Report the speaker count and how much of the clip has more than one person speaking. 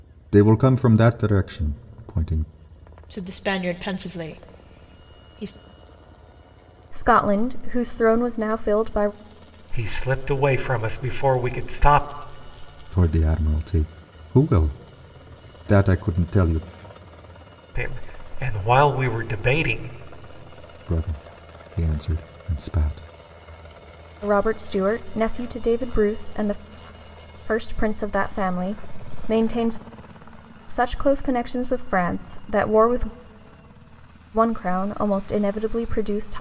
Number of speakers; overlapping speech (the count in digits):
4, no overlap